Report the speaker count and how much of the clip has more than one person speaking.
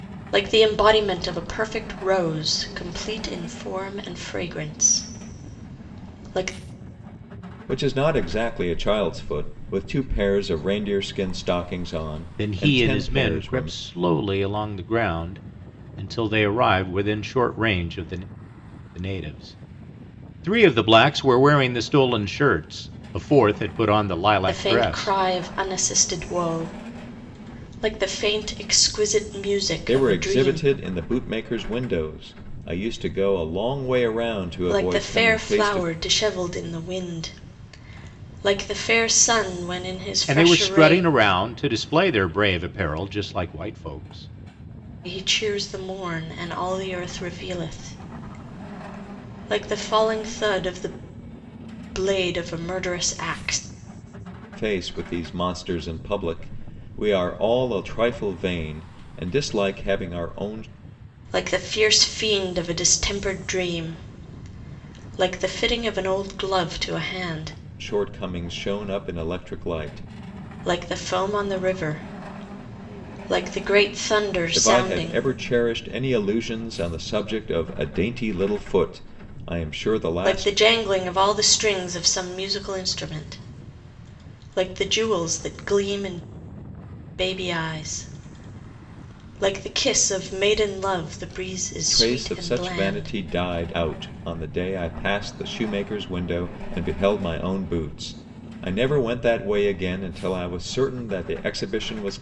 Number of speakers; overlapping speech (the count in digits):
3, about 7%